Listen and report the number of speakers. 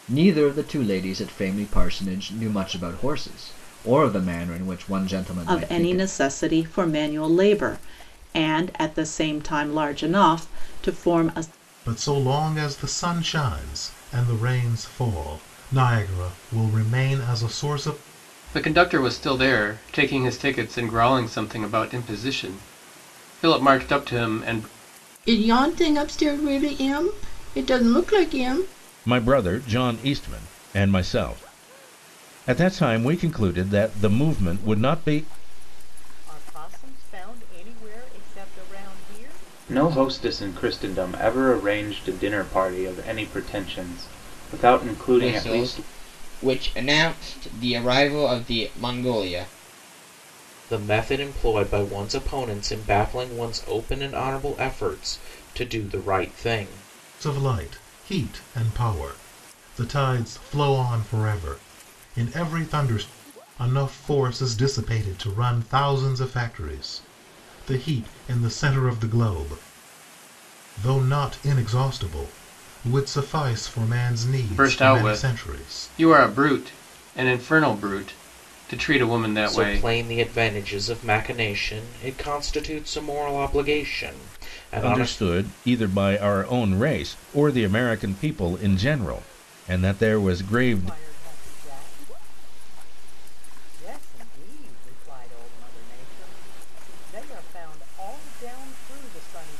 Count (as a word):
ten